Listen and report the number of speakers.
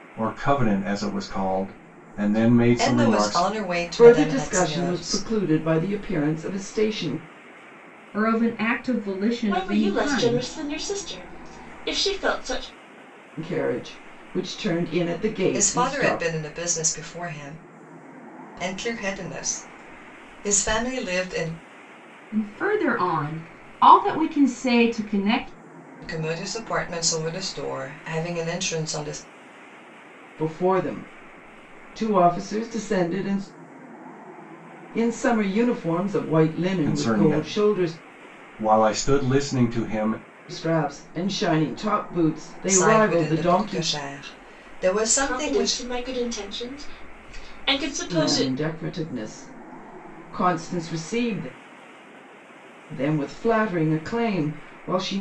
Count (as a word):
five